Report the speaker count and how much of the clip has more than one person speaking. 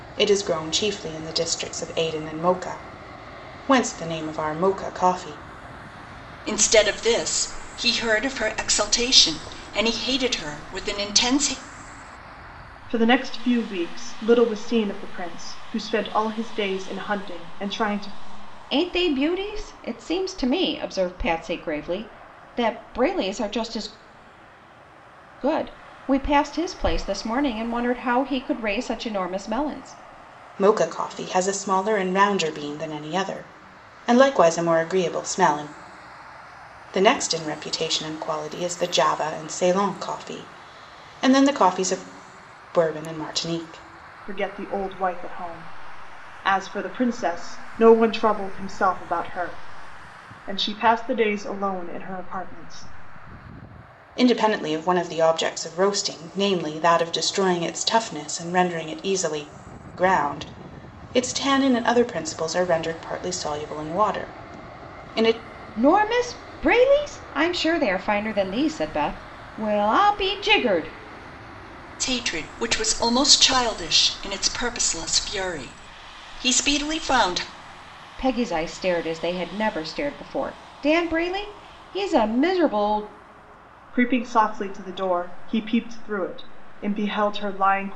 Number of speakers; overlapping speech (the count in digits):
4, no overlap